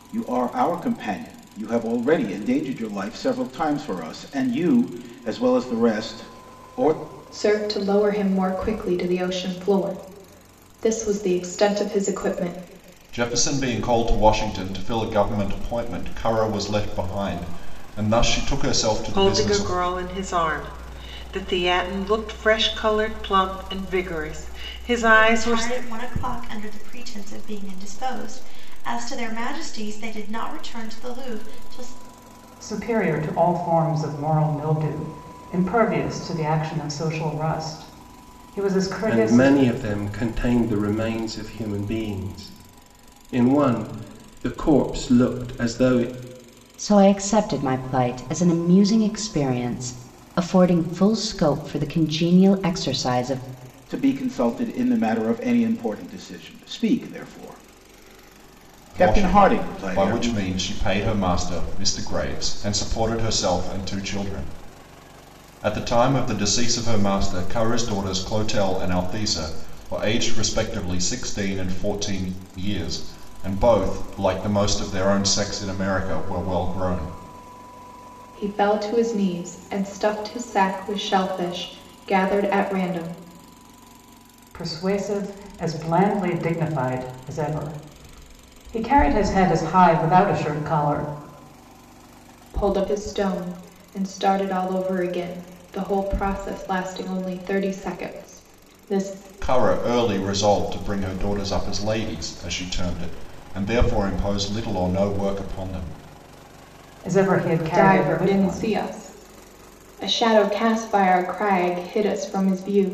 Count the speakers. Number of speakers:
eight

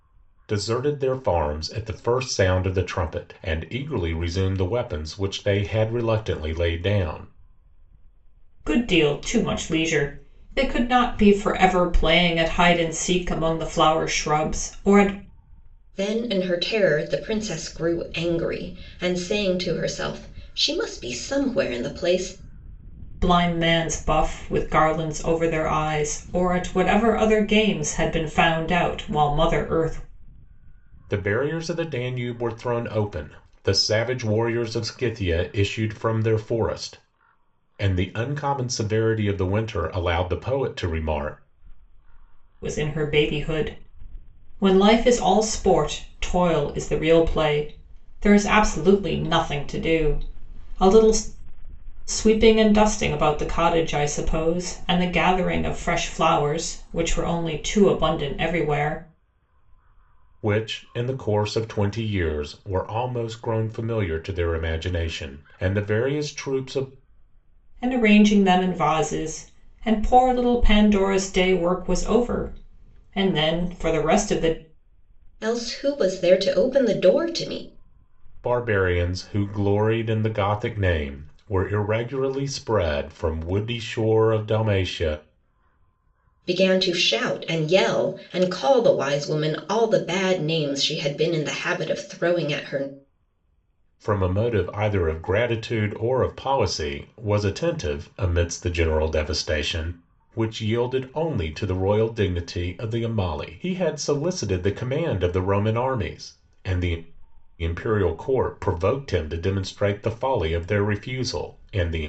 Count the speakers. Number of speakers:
three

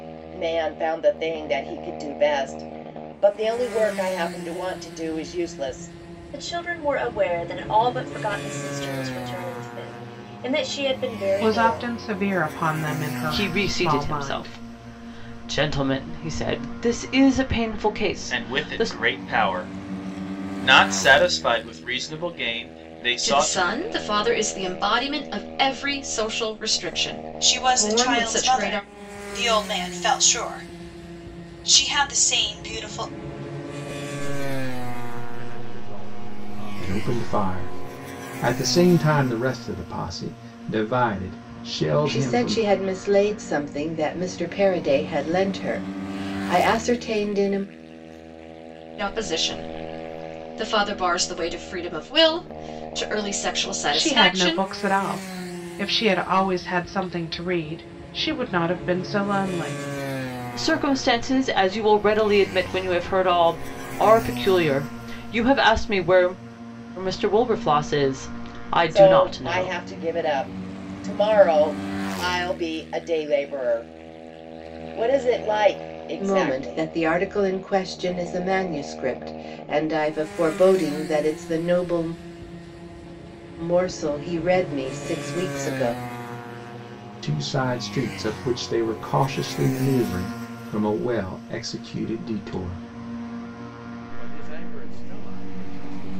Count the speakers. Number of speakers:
ten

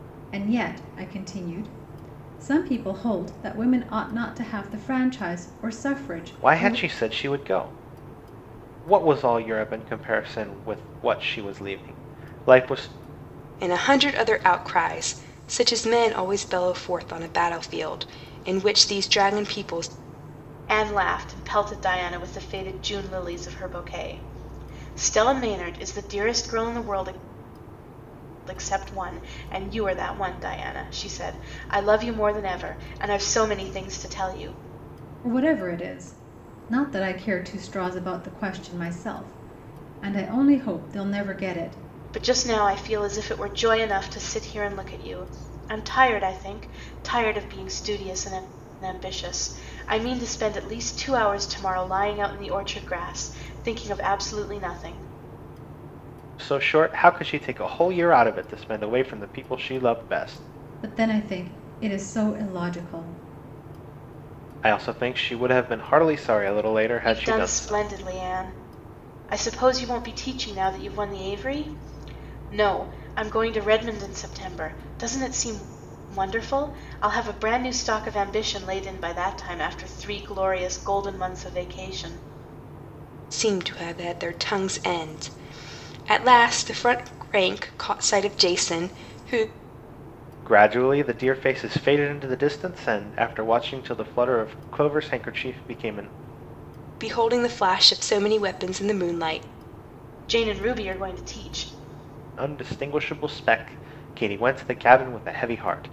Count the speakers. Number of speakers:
four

